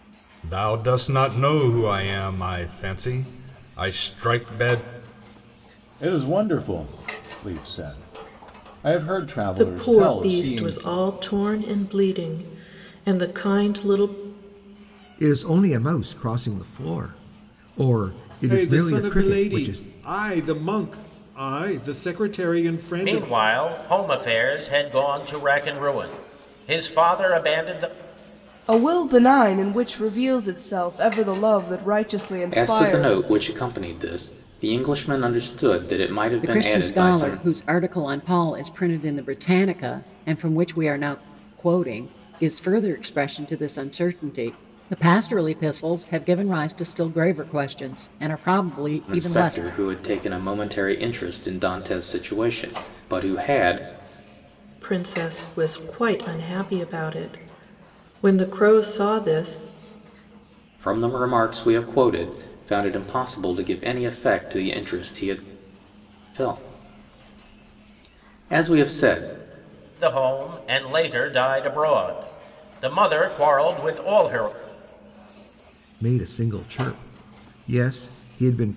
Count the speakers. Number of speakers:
9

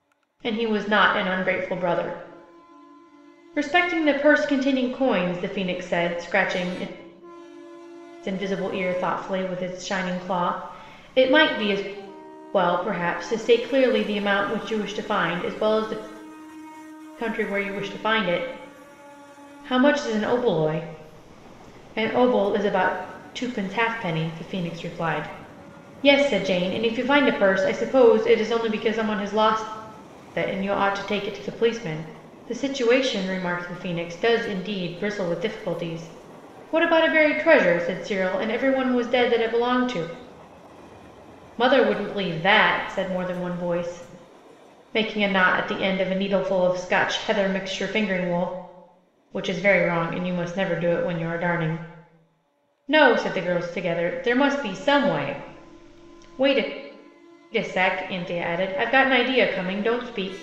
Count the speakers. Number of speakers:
1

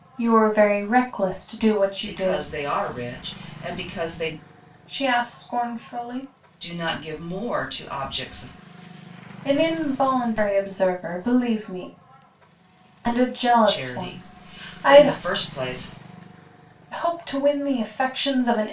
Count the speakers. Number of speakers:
2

